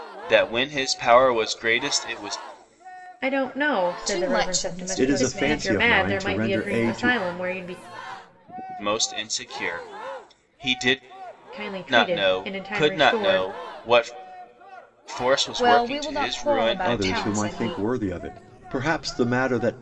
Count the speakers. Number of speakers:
four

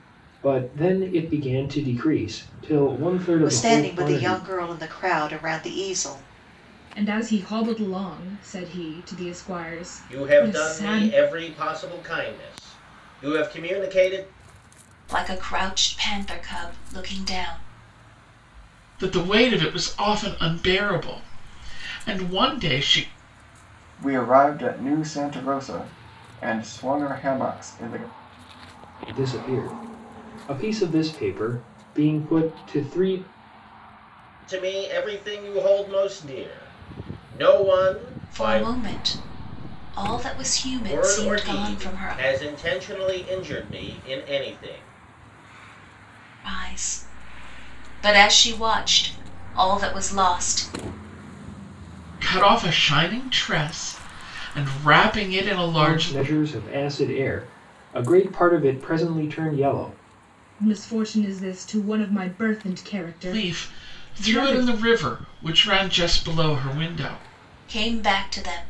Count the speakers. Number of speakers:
seven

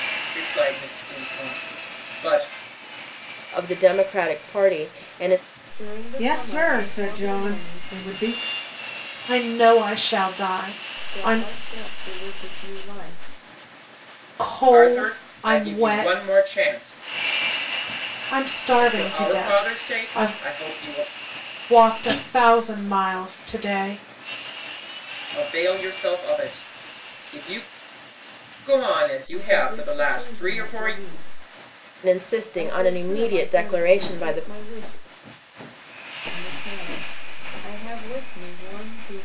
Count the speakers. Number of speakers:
five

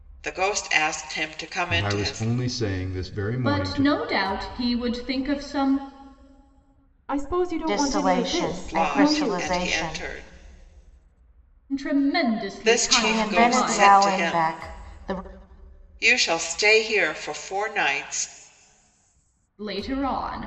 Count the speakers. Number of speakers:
five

